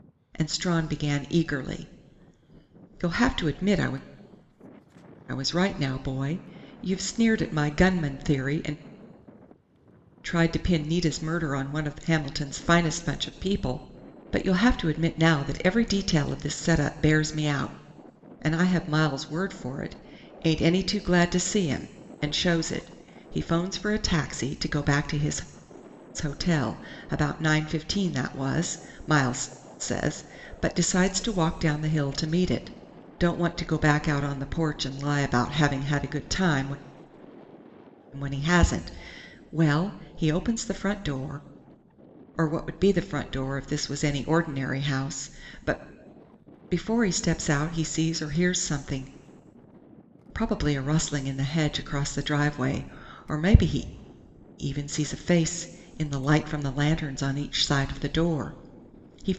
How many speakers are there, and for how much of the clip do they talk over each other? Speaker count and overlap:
1, no overlap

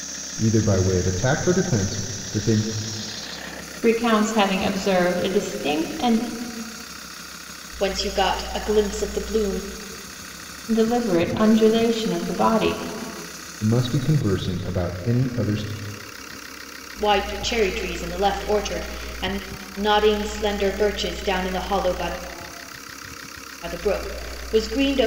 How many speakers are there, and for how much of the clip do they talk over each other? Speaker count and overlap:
3, no overlap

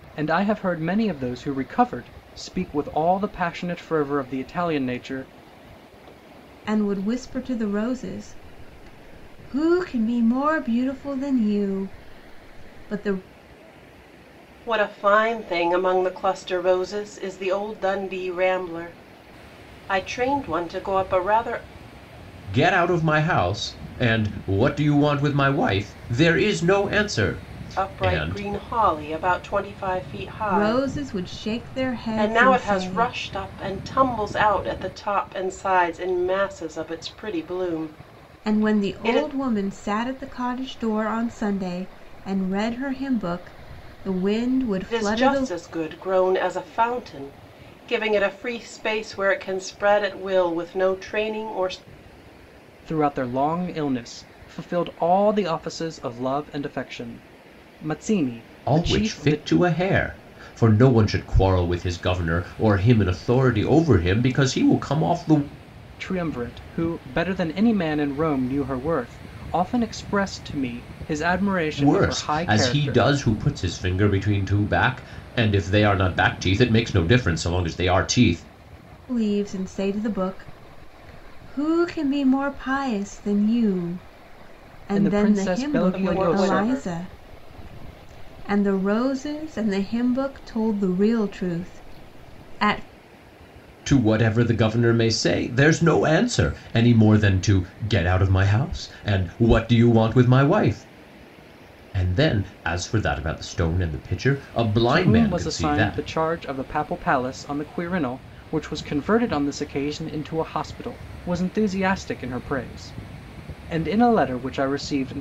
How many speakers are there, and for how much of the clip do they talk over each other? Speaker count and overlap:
4, about 8%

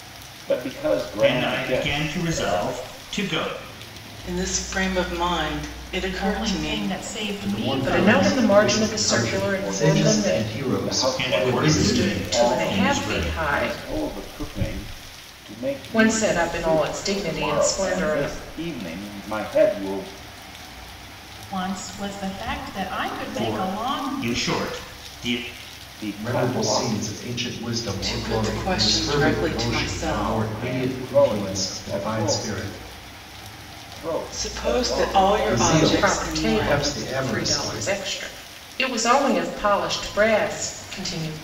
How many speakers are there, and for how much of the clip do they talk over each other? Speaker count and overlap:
6, about 51%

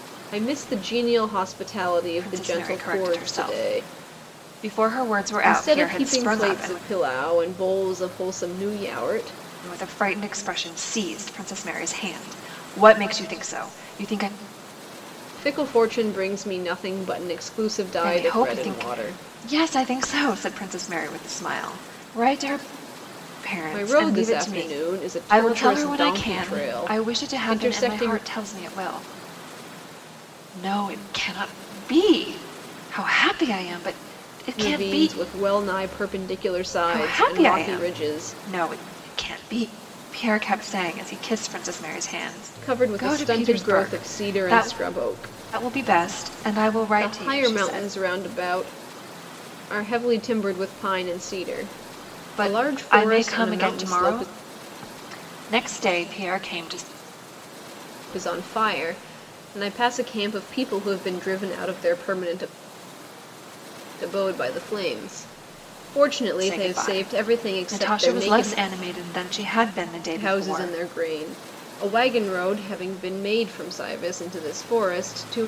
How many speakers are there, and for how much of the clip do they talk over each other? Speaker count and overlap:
2, about 26%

